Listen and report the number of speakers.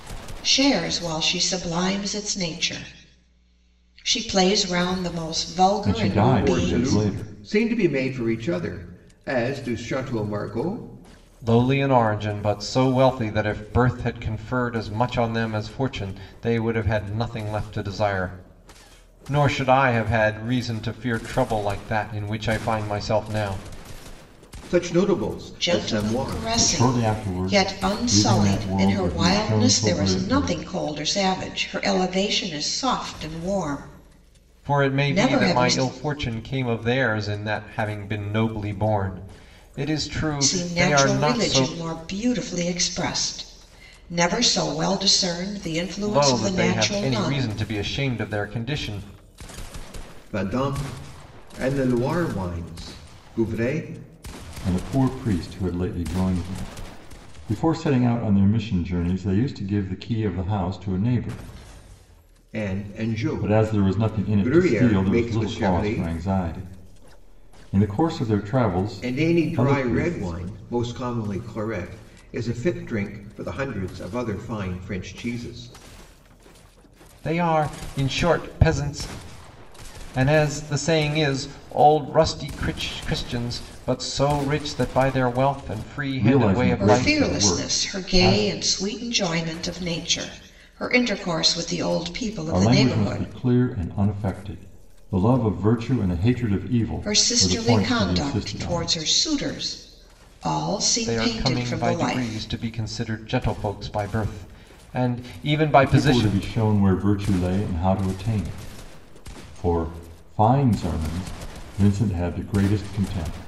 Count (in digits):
4